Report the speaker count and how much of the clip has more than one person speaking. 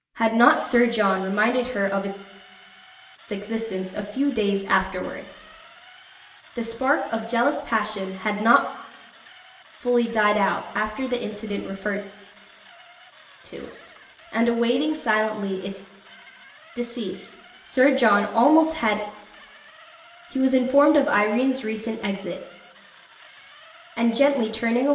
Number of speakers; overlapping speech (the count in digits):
1, no overlap